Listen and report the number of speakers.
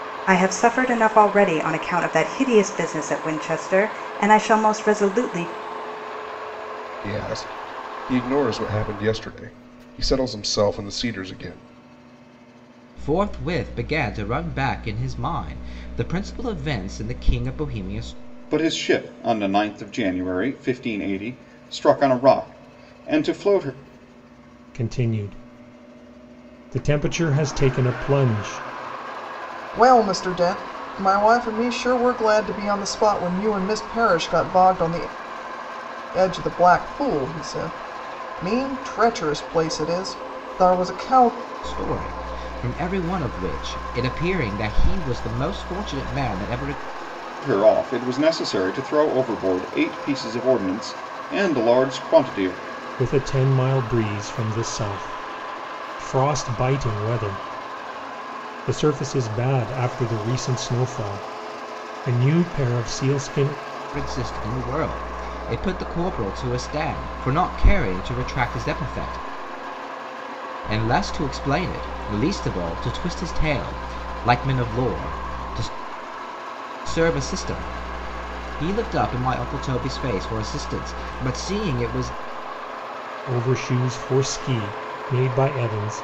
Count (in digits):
6